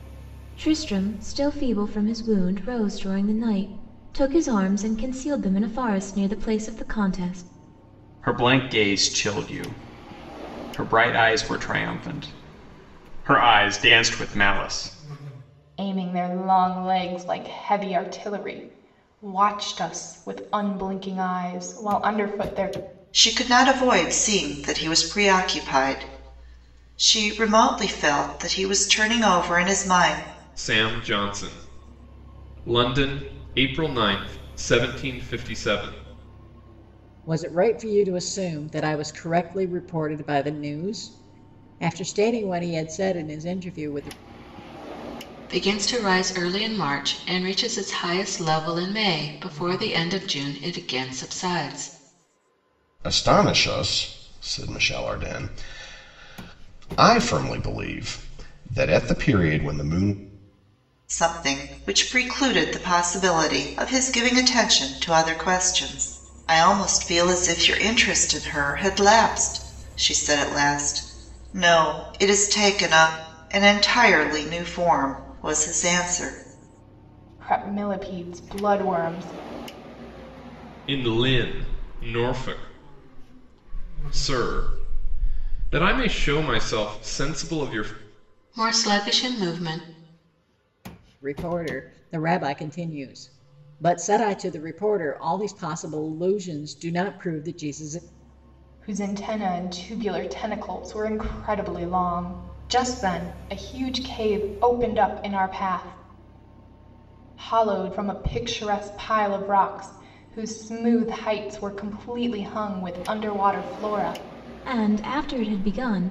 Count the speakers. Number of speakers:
8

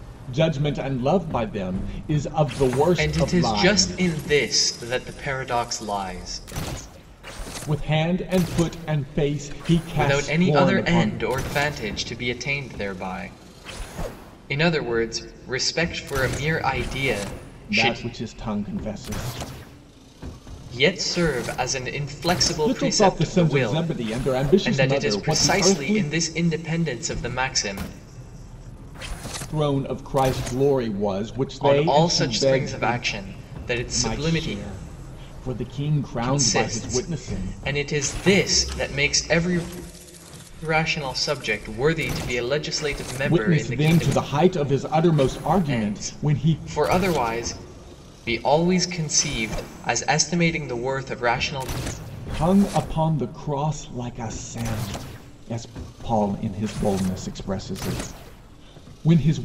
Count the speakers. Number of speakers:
2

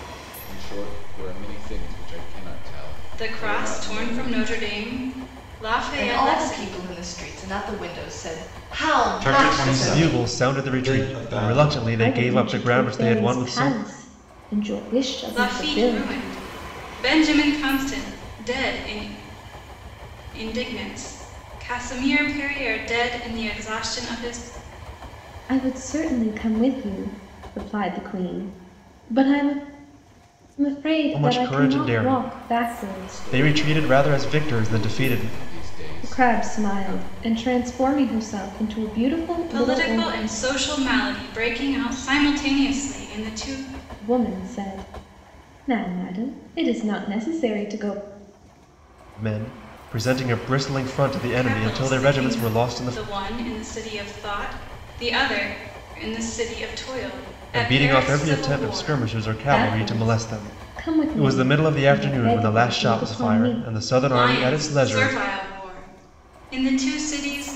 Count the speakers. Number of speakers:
6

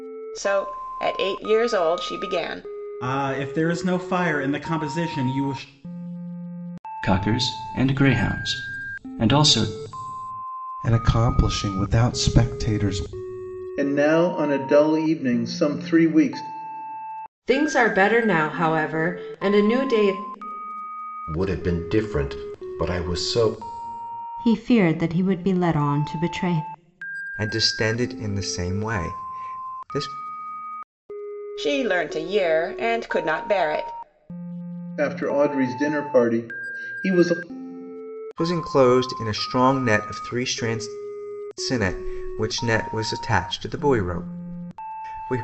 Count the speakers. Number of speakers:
9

